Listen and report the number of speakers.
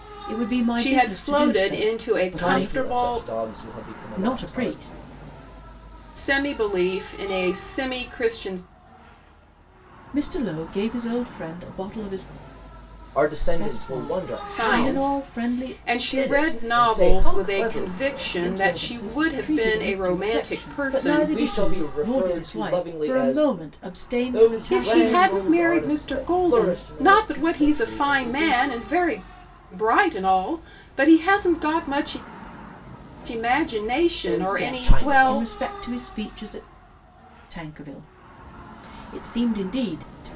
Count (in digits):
3